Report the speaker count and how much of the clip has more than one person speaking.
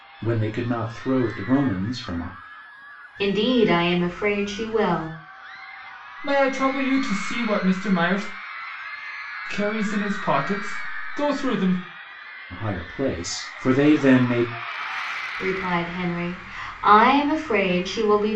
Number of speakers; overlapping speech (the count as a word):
three, no overlap